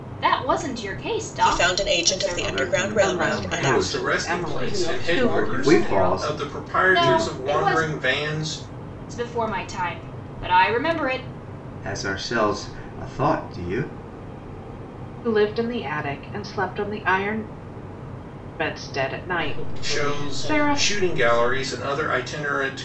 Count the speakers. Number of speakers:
six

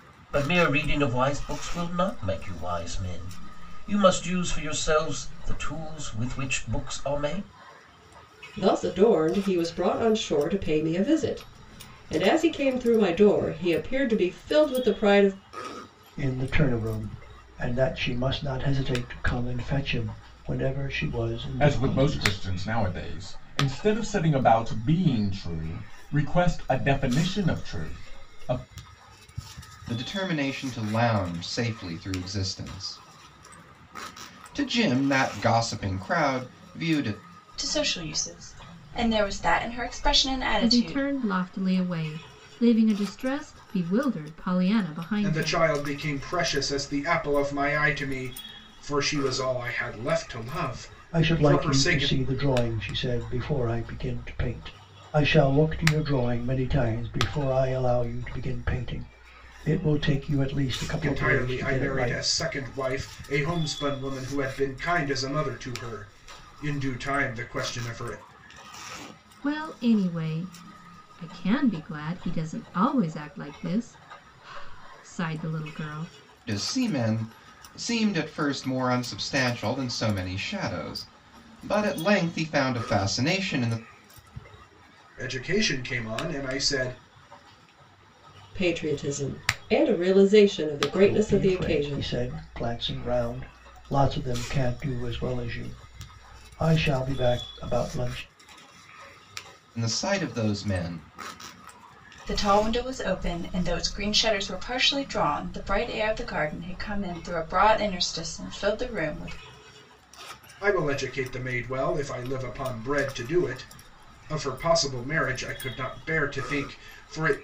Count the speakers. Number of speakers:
eight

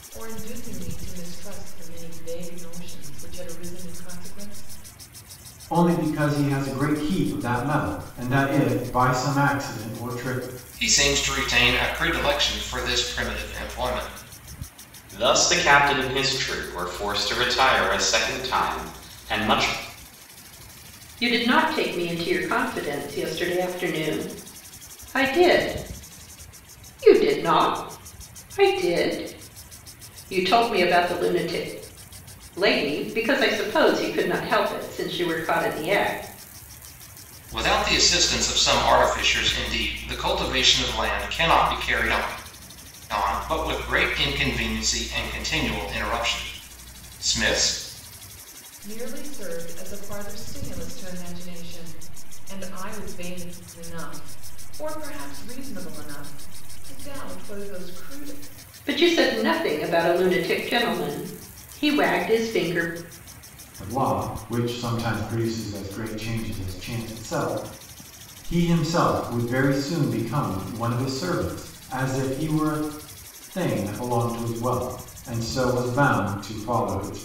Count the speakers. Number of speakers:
five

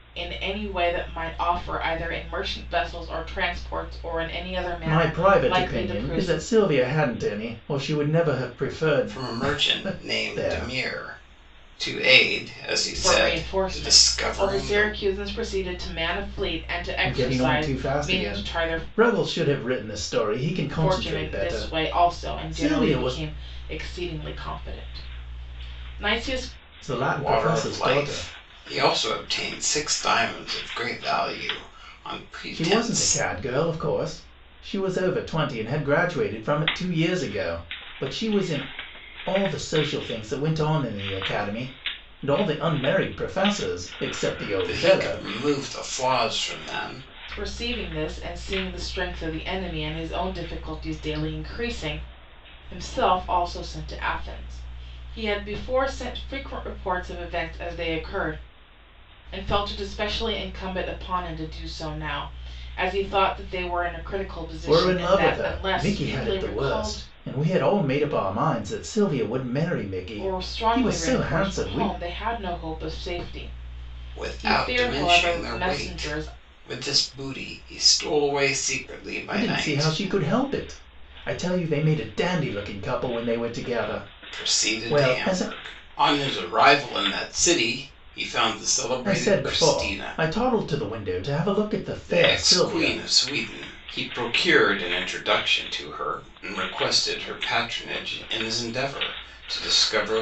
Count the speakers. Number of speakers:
three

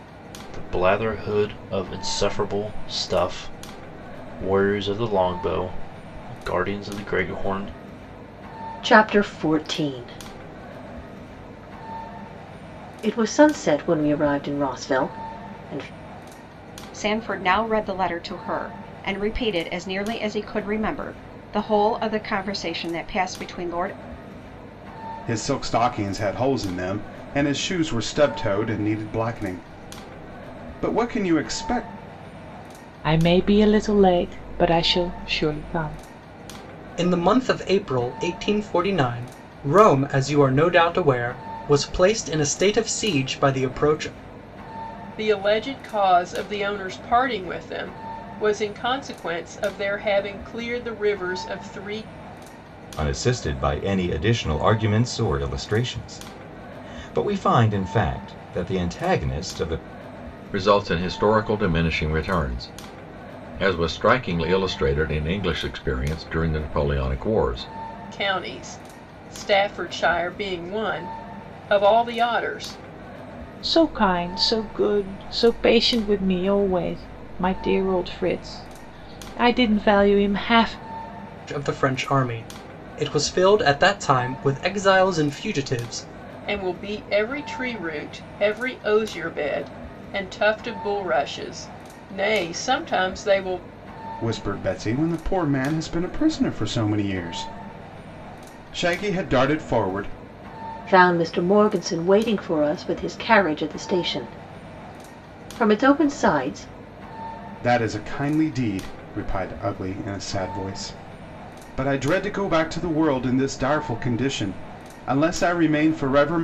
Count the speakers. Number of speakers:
nine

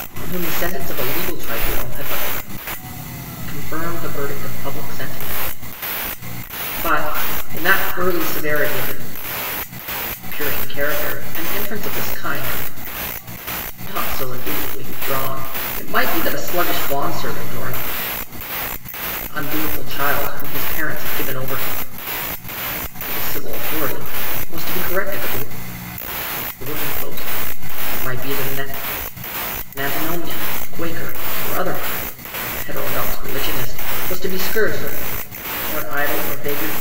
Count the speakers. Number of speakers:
one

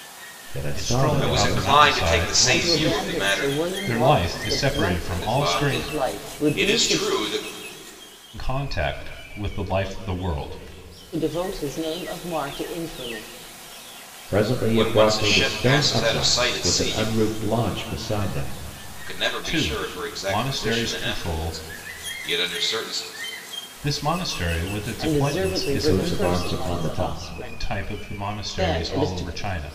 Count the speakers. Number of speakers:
four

